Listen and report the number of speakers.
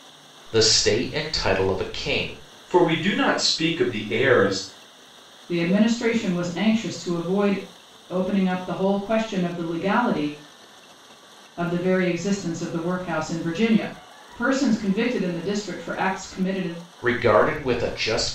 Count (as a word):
three